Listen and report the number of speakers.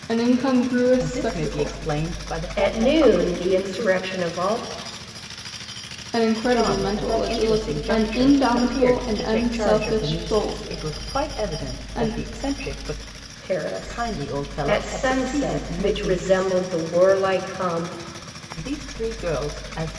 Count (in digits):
3